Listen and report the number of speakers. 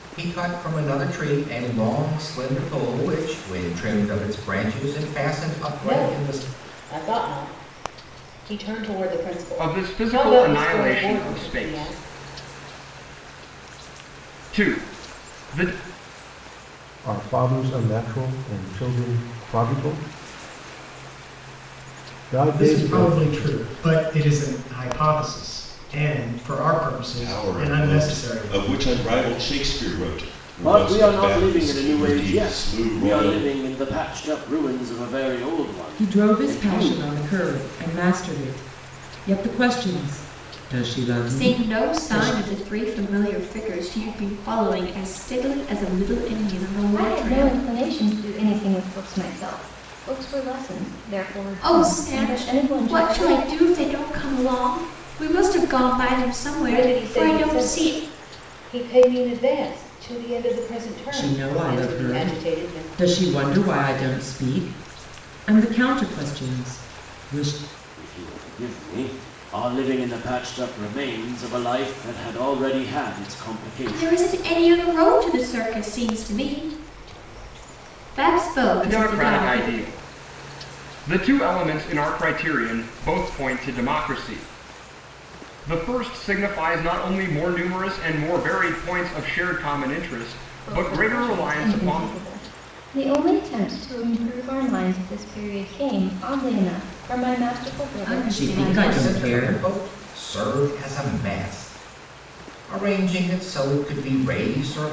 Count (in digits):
10